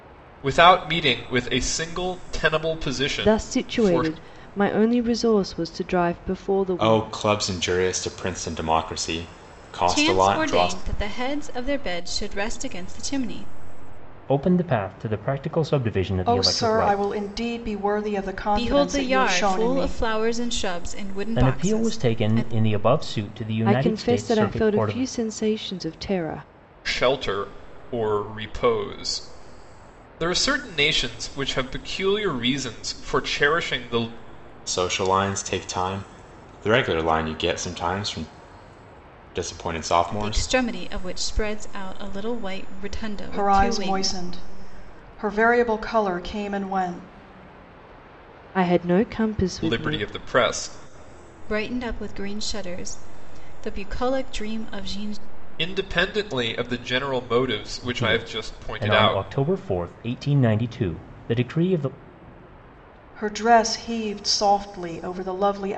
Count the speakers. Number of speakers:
6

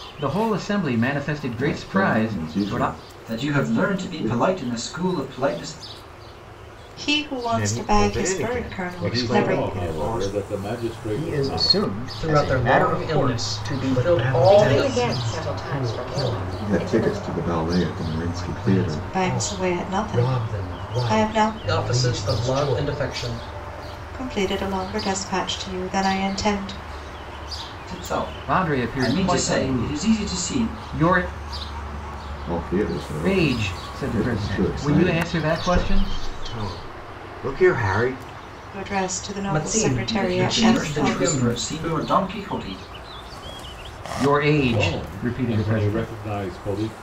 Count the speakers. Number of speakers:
10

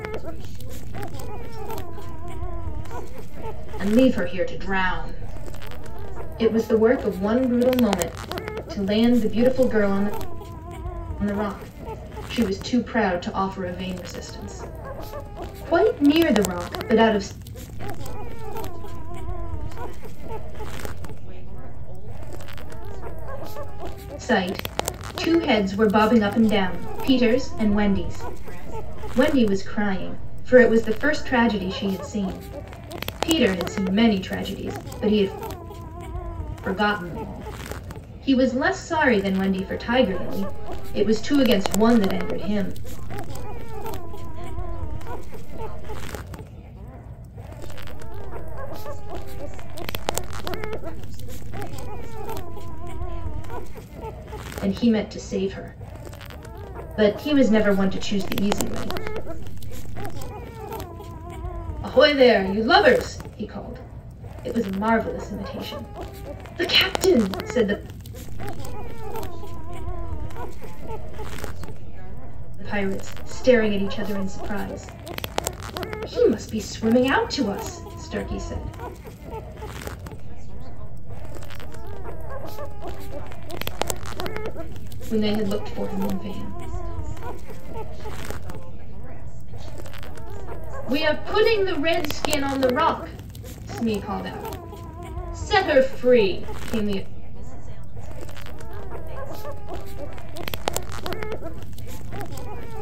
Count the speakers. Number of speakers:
2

